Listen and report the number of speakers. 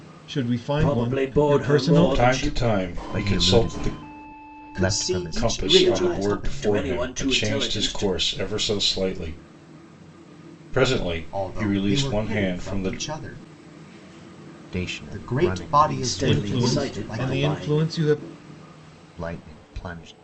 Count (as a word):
five